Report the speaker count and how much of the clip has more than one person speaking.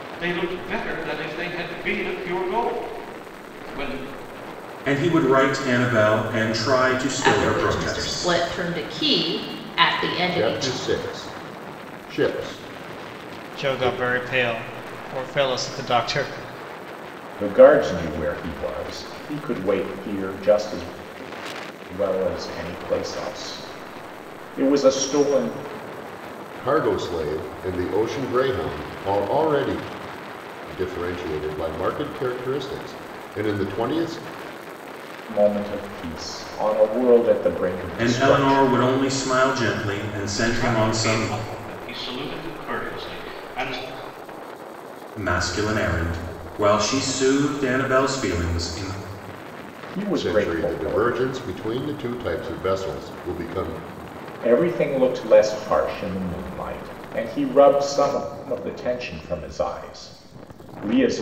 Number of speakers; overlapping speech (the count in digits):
6, about 8%